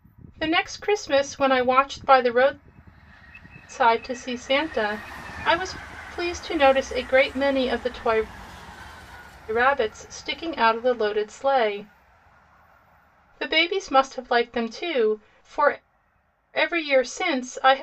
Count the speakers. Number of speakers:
1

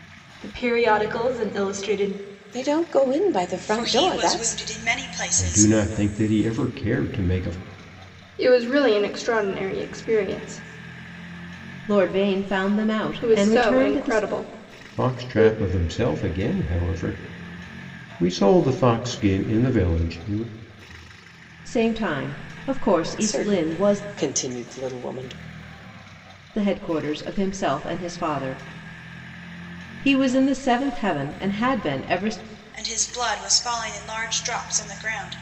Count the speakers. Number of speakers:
6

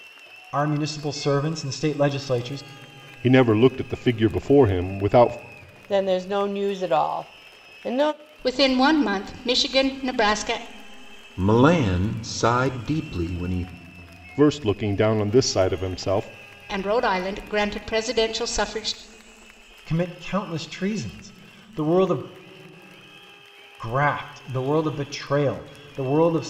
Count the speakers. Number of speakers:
5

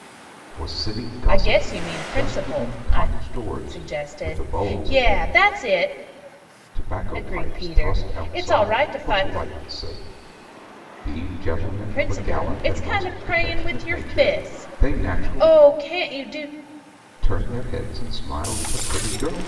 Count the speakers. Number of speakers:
2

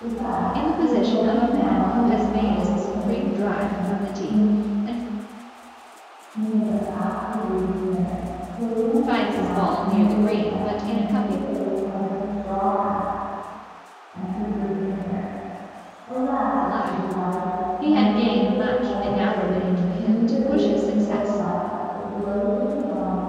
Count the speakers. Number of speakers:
2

